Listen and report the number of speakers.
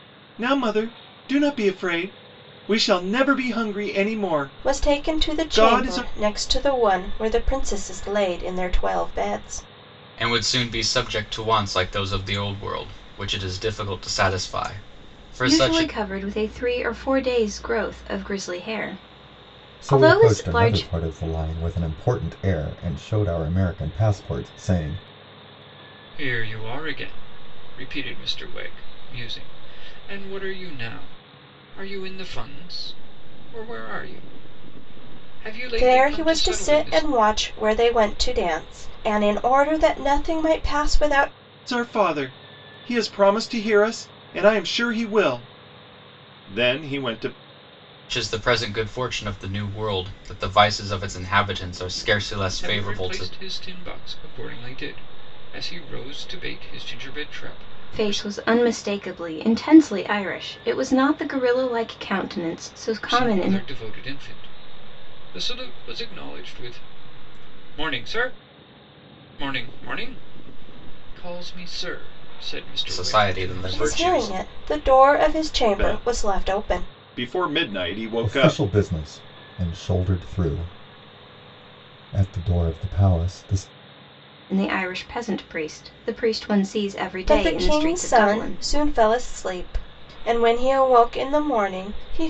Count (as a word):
six